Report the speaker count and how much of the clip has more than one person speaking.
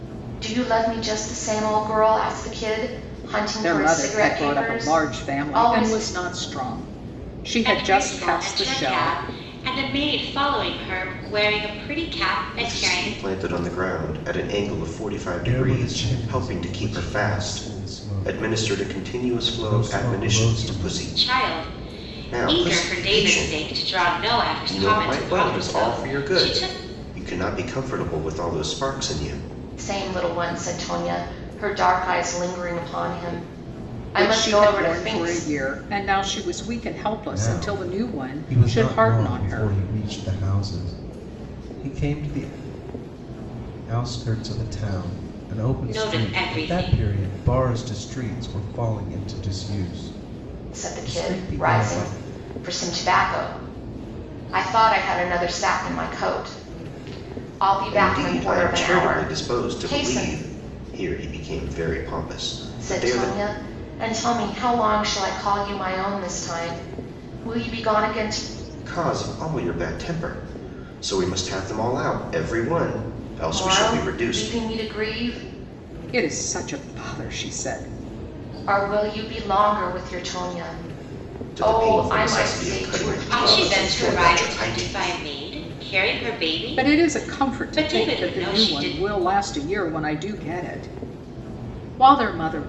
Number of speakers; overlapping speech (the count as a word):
five, about 34%